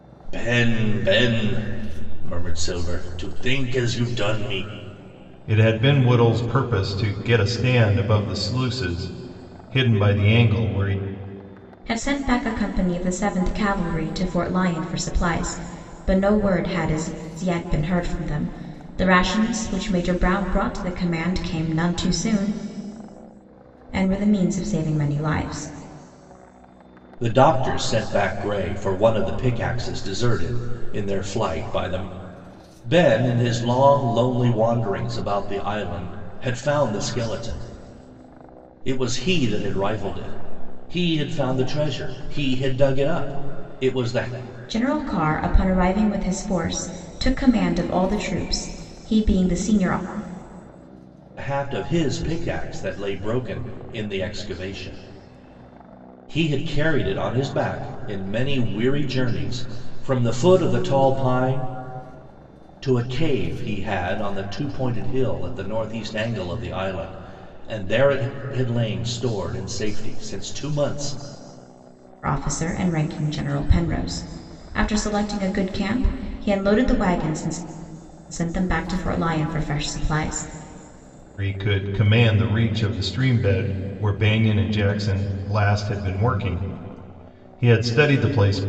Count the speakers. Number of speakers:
3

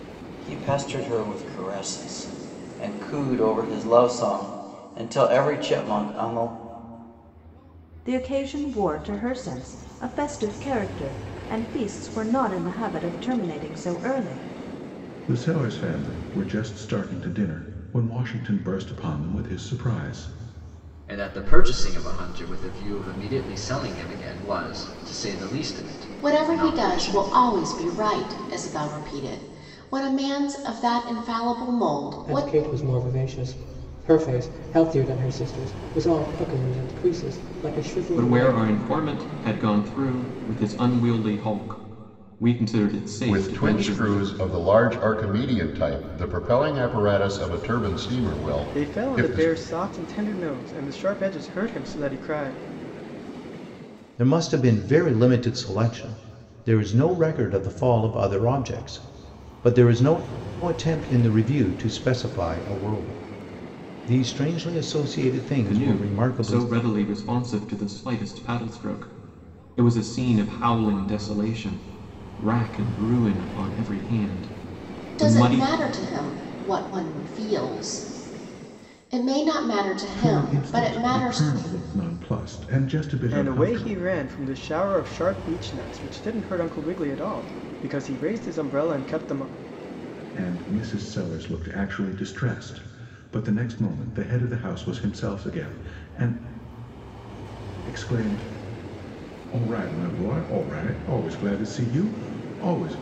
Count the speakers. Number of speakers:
10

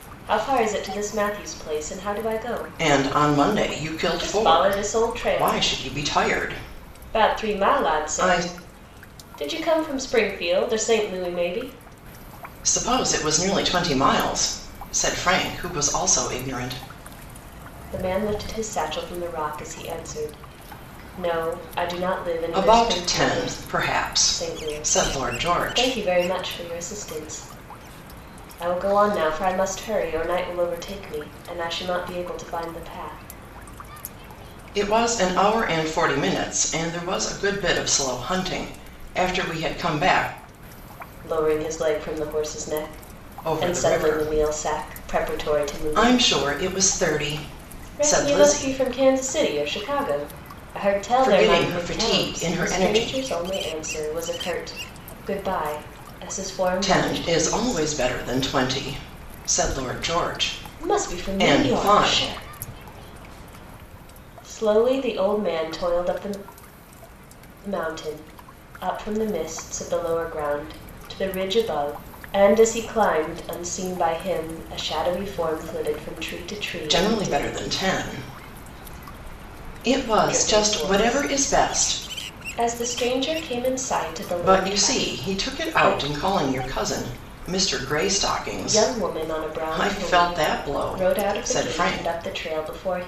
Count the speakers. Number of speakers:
2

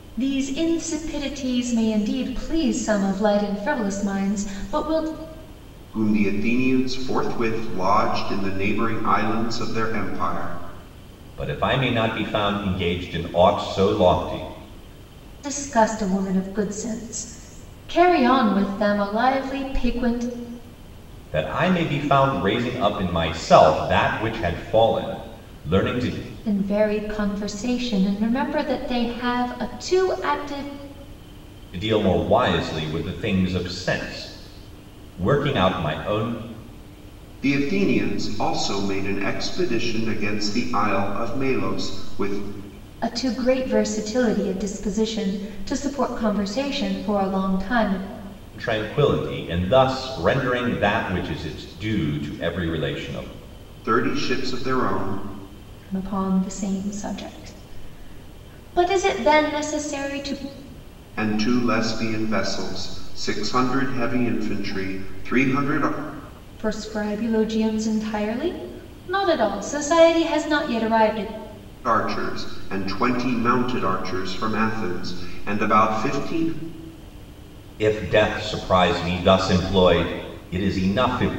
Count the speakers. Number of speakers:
3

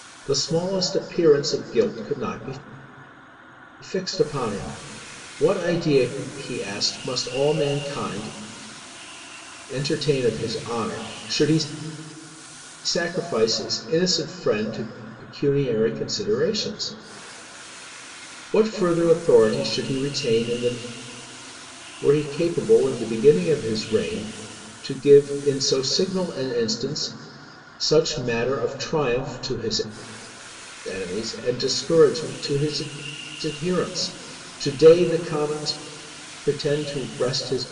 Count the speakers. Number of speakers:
1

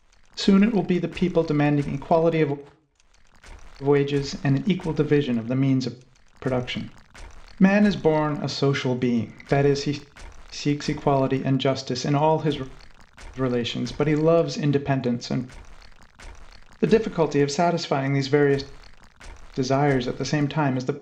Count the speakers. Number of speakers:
1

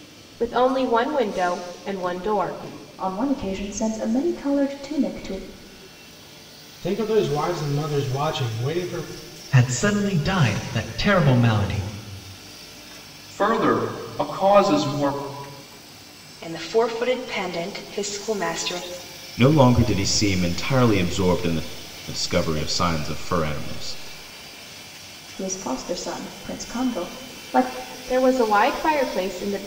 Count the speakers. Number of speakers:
7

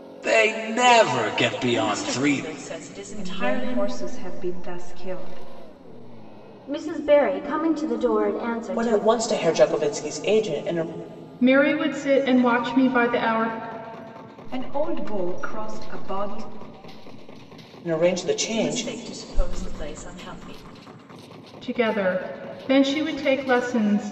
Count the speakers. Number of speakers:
6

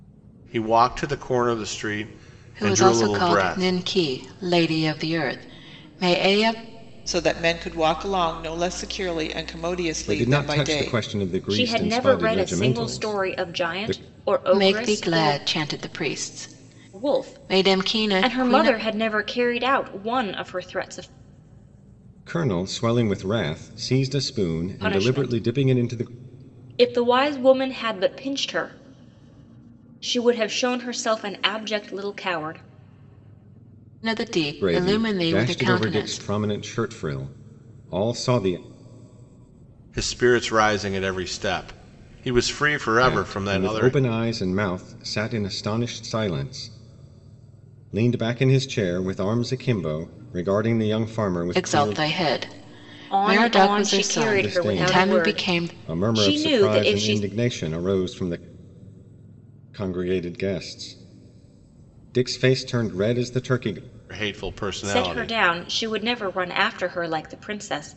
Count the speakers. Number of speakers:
5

